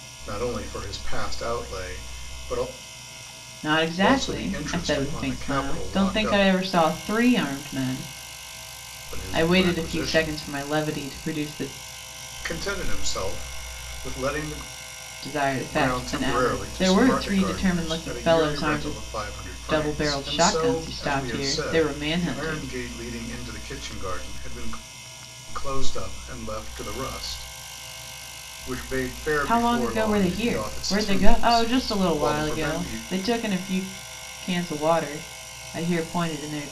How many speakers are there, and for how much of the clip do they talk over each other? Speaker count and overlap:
two, about 37%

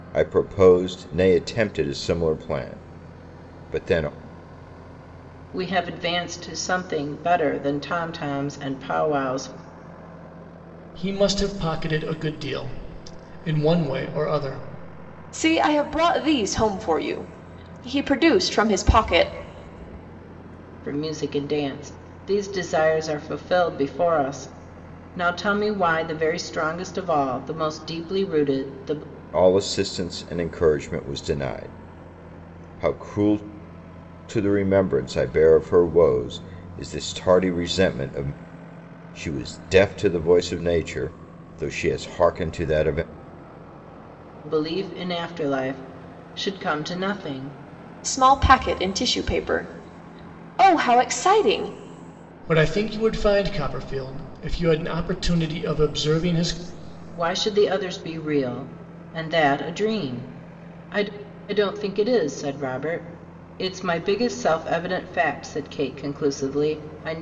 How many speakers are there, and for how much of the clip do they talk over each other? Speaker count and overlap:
four, no overlap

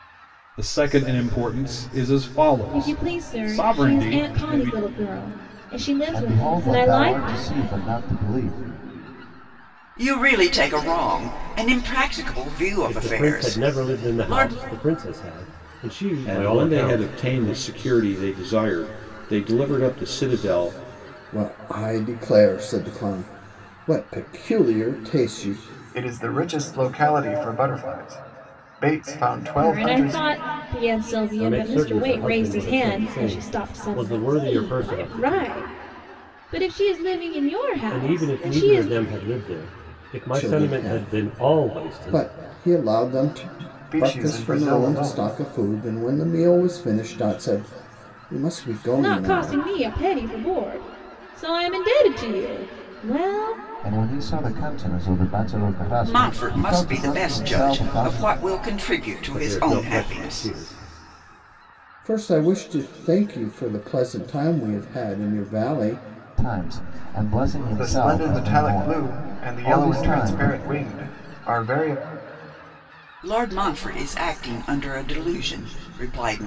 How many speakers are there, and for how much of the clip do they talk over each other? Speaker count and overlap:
eight, about 30%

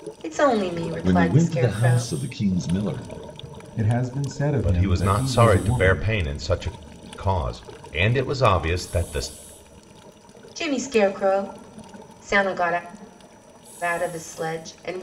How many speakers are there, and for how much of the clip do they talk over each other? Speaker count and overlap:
four, about 18%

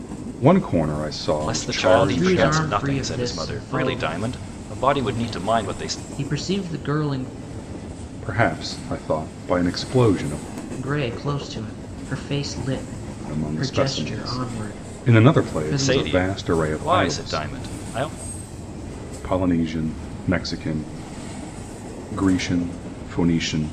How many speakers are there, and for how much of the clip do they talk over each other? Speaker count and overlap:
three, about 30%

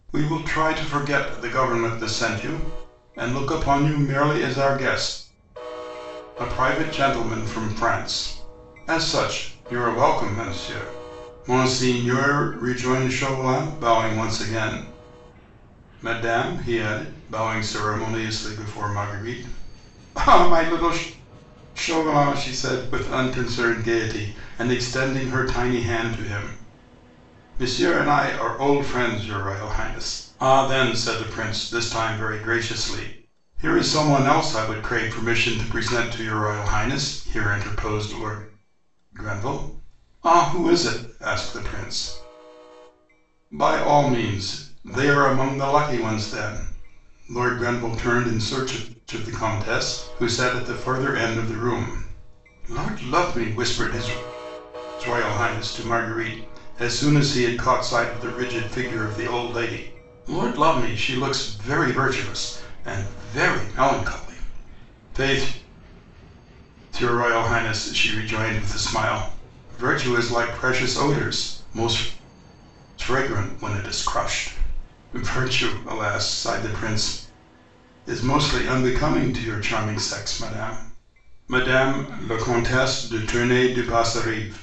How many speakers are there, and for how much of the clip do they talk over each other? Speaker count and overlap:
one, no overlap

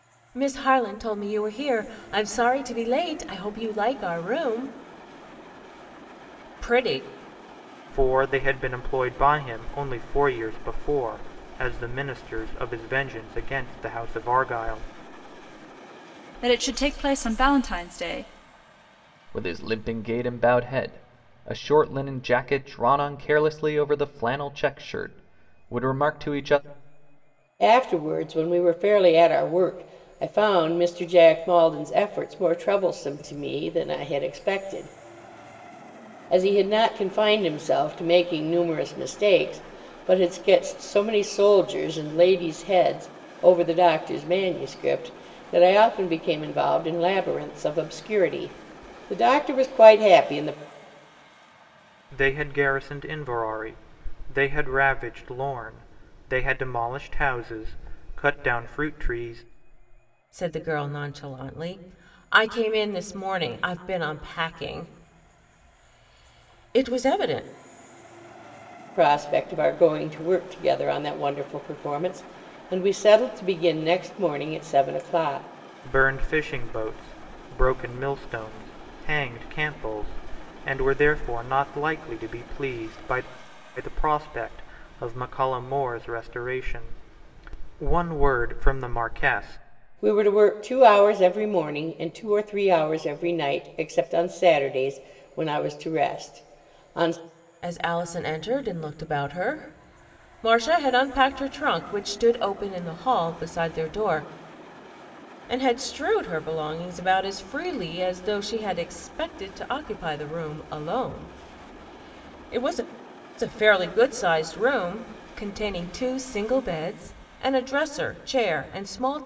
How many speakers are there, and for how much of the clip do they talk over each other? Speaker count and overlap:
five, no overlap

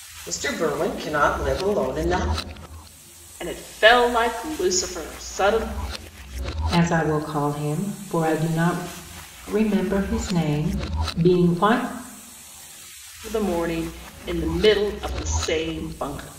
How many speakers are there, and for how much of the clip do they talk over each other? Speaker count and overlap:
three, no overlap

